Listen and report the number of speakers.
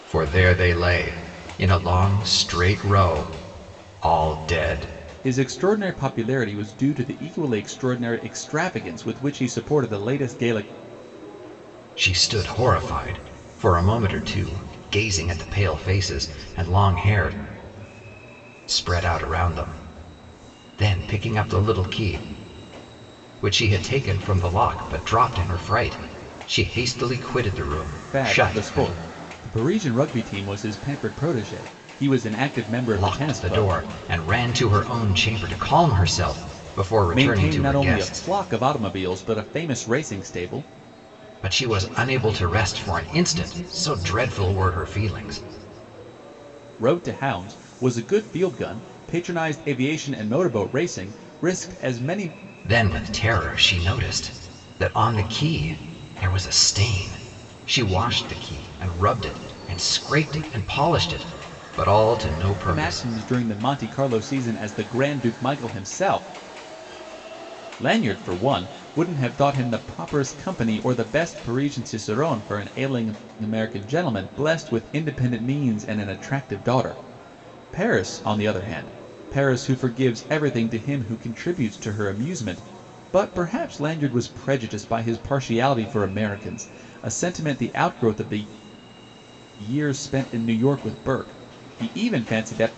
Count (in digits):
2